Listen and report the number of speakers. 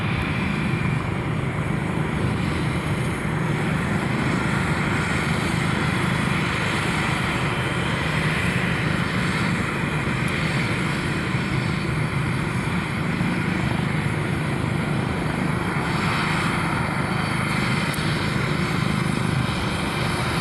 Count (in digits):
0